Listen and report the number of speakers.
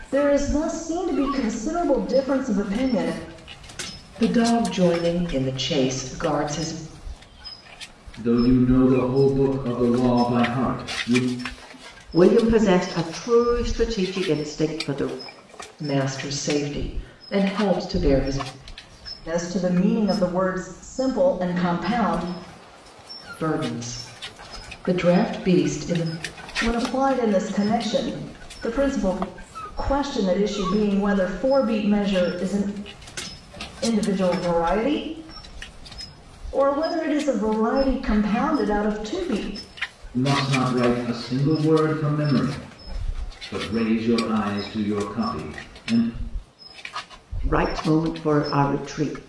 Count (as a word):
four